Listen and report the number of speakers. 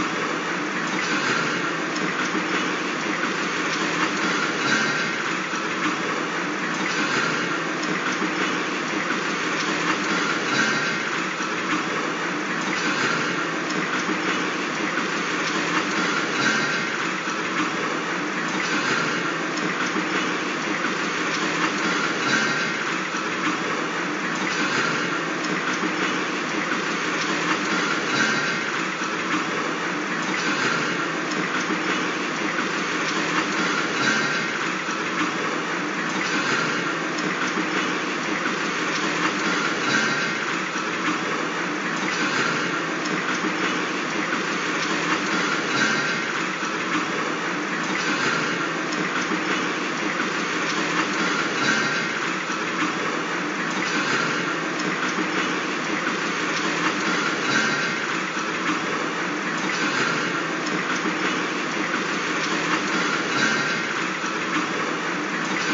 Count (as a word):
zero